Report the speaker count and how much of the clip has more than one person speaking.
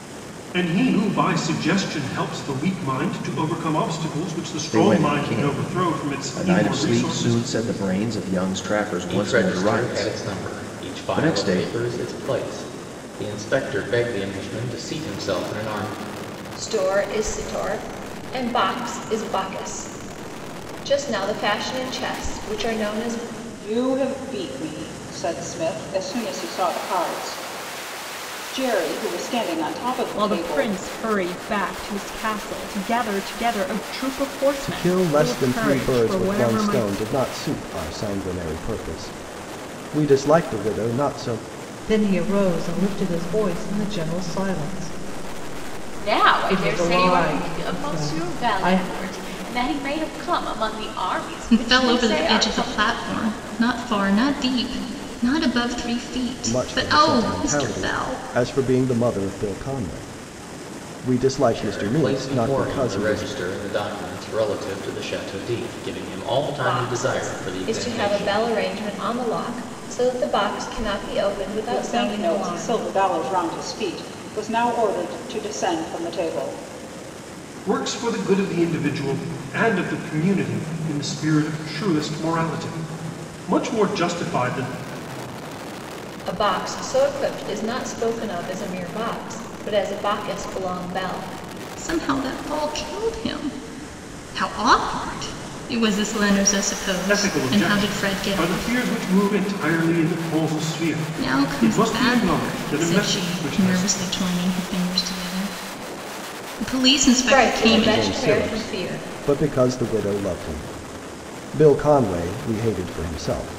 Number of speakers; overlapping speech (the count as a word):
ten, about 23%